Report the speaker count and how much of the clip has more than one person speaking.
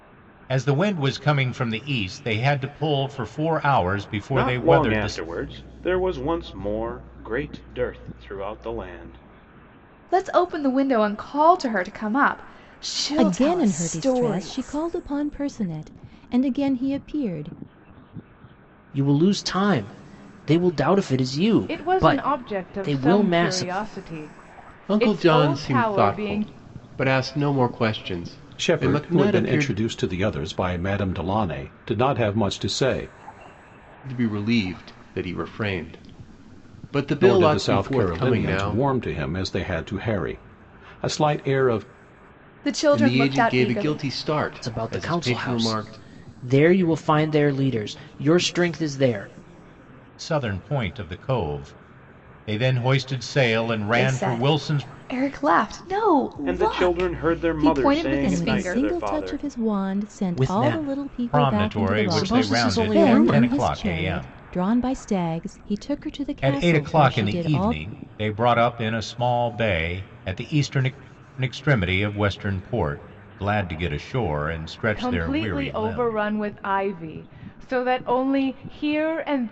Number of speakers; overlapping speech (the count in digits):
8, about 29%